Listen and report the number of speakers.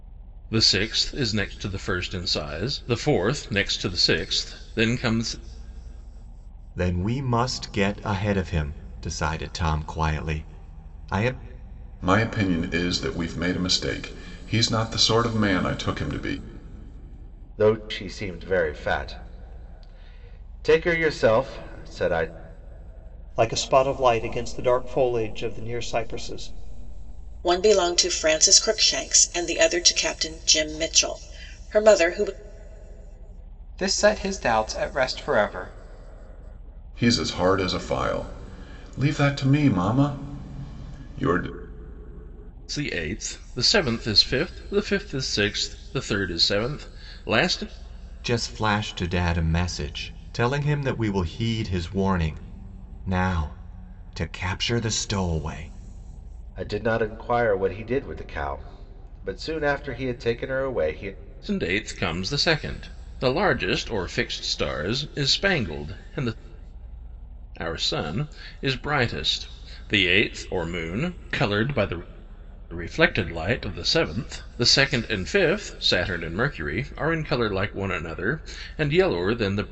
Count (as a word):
seven